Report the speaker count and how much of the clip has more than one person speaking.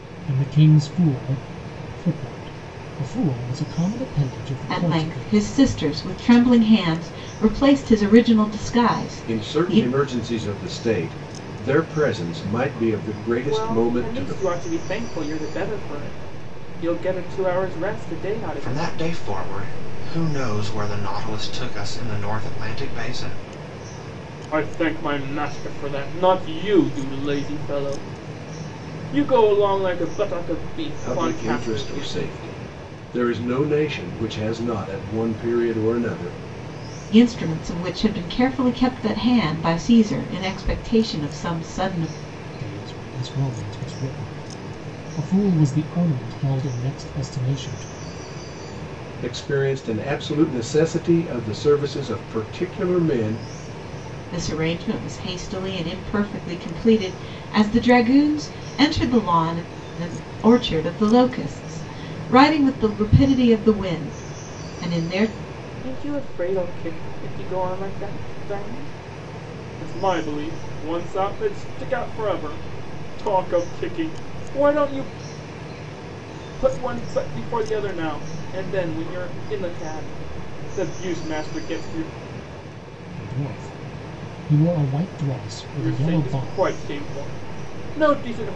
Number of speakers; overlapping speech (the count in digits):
5, about 6%